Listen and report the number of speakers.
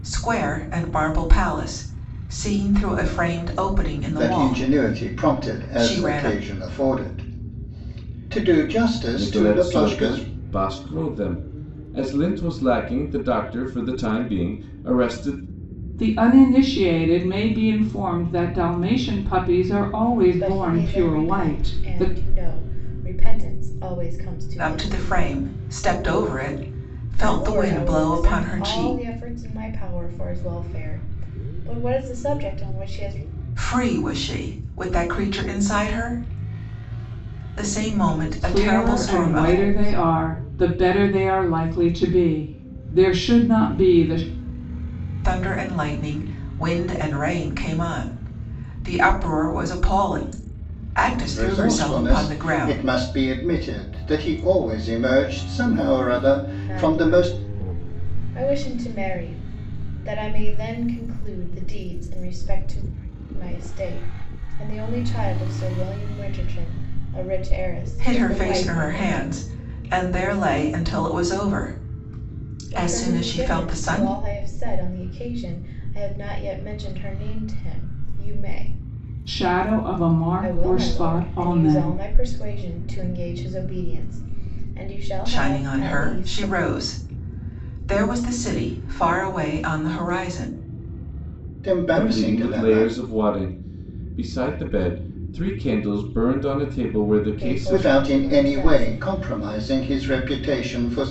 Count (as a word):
five